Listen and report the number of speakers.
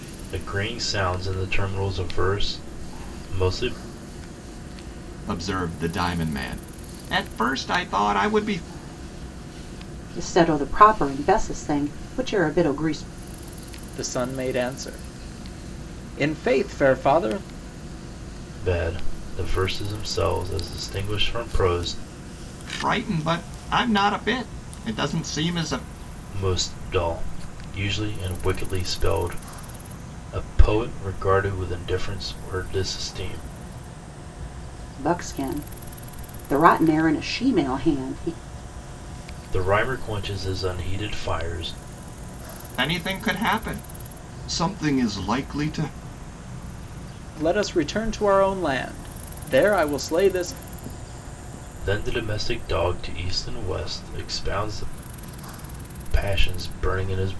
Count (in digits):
4